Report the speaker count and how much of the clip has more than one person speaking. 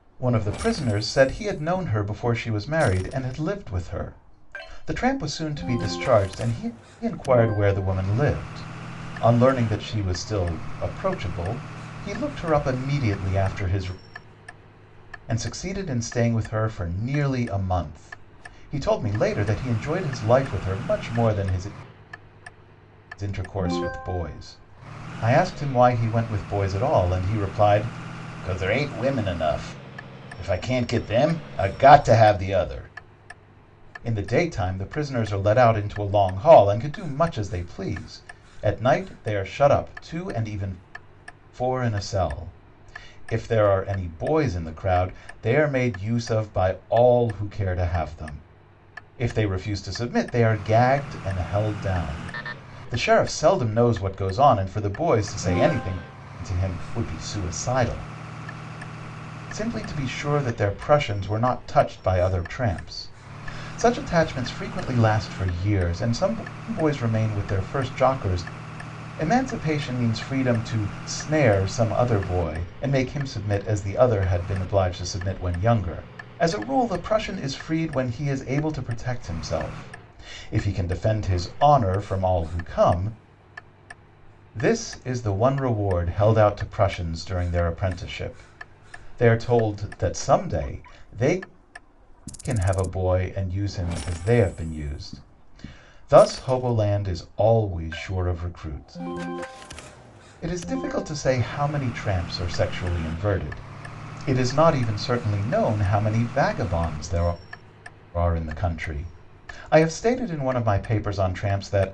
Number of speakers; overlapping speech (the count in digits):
1, no overlap